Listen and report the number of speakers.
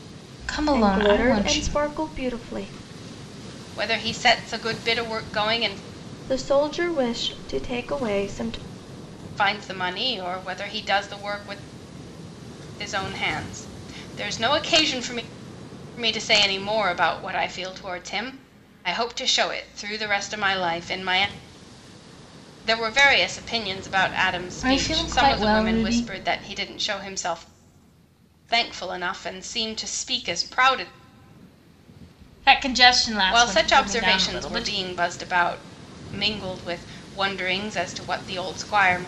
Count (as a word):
three